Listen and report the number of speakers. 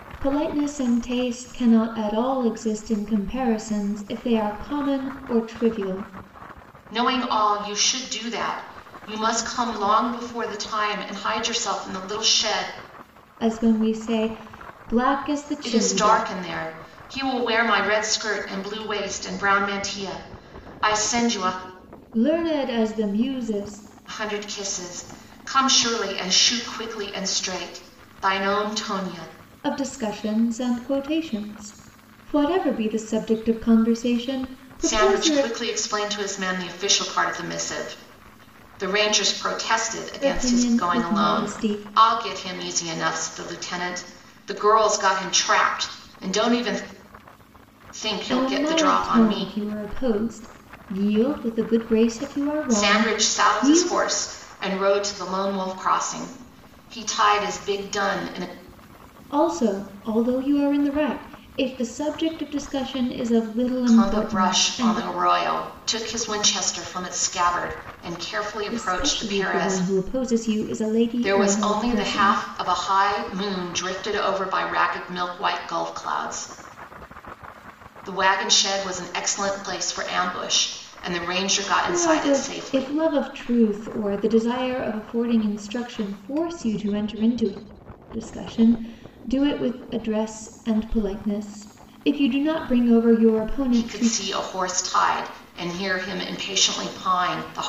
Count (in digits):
2